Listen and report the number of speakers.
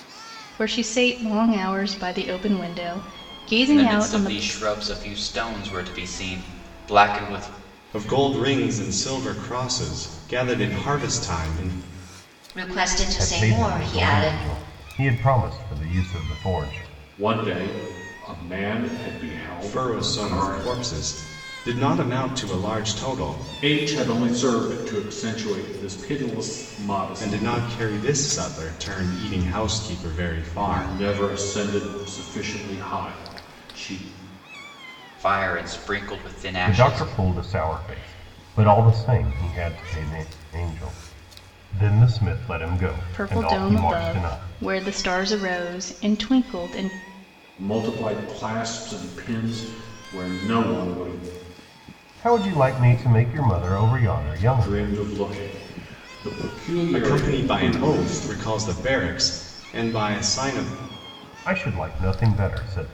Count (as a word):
six